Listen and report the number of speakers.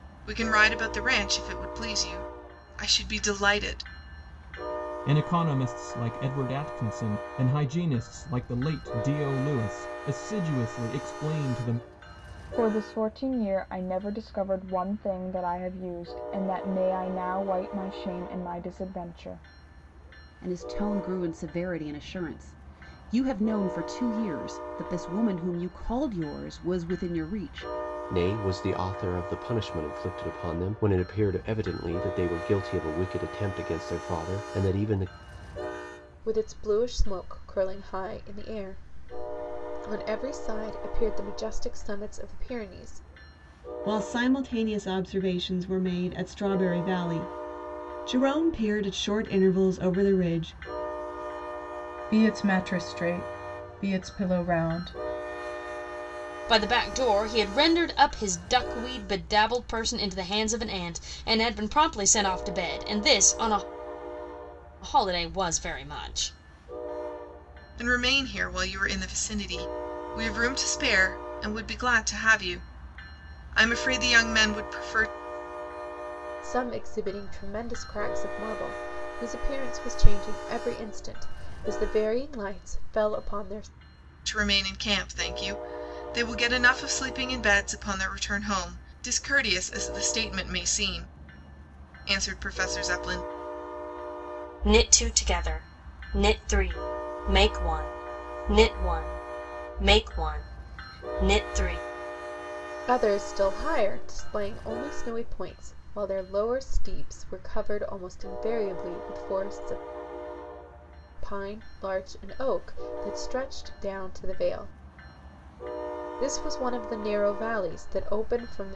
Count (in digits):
9